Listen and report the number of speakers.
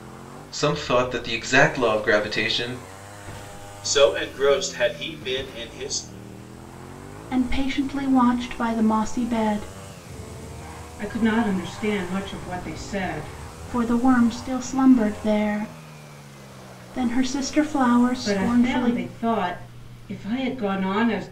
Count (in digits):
4